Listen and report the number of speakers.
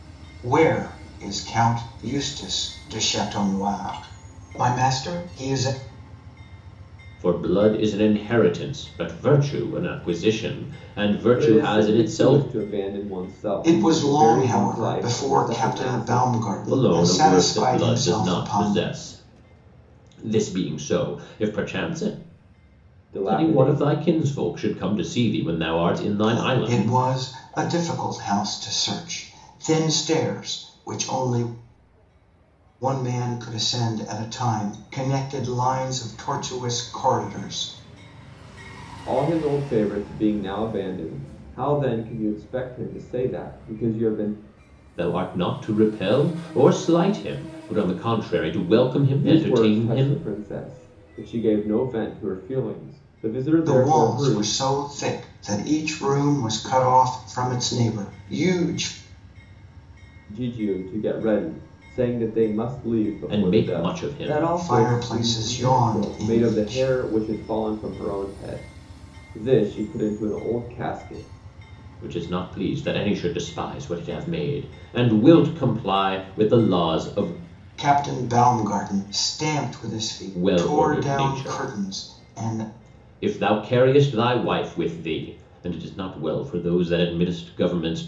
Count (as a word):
three